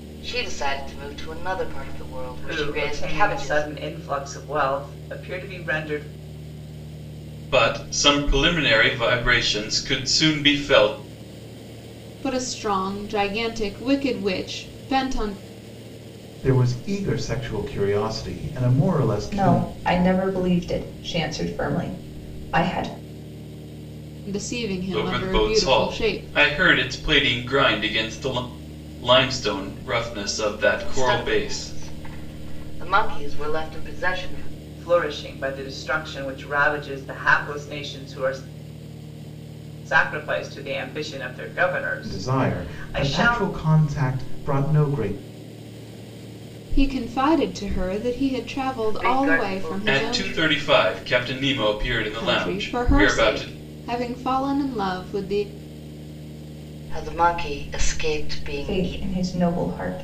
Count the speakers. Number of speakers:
6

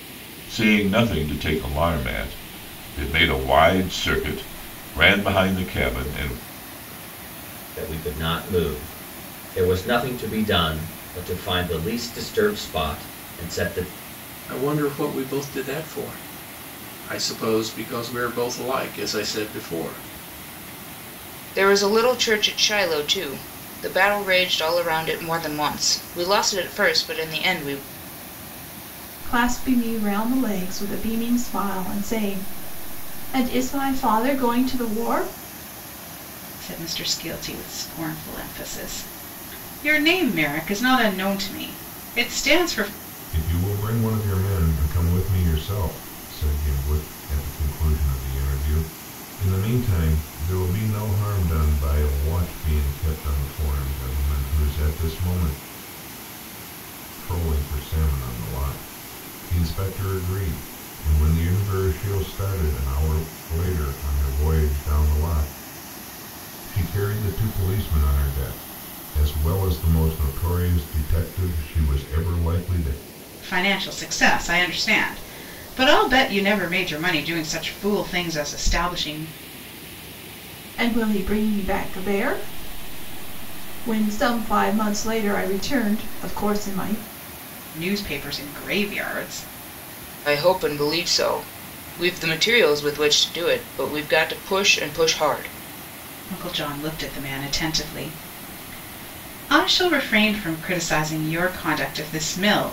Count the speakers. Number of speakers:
7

